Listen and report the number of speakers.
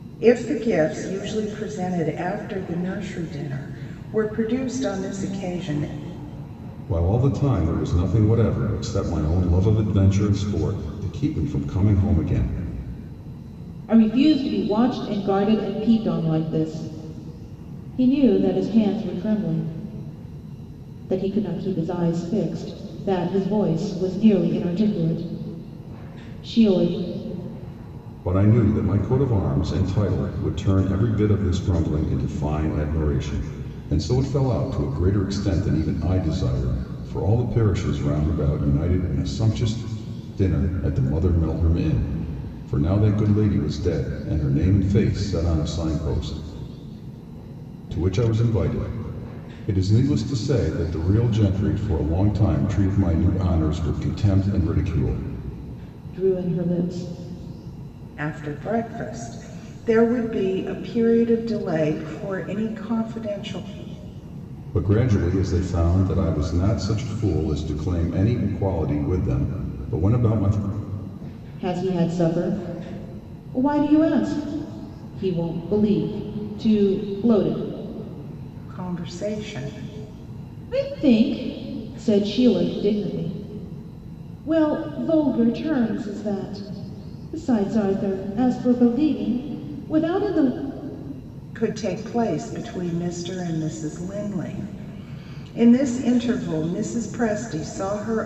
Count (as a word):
three